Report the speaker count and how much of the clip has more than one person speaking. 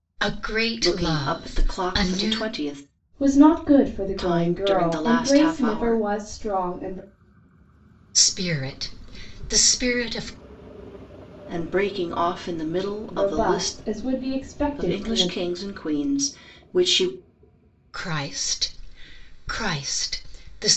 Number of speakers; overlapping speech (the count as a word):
three, about 24%